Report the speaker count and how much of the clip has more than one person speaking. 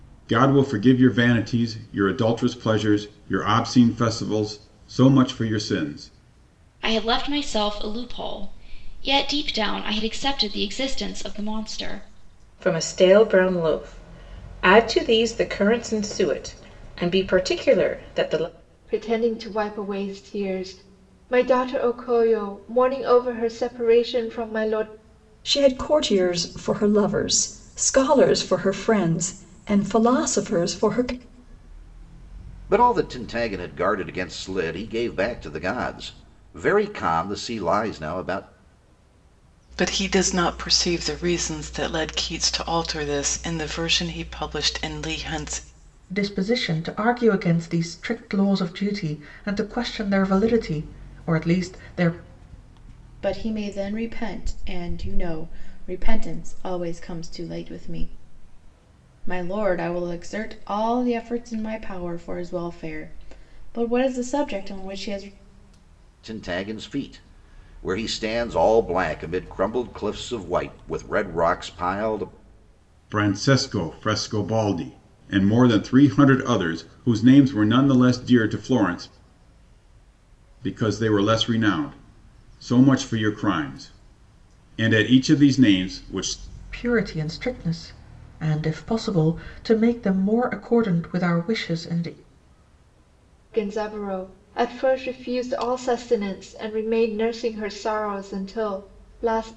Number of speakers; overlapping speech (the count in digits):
9, no overlap